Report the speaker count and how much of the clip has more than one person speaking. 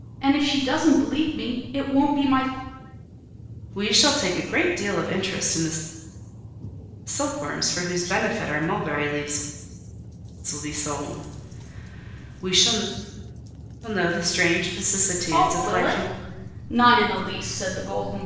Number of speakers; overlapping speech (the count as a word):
two, about 5%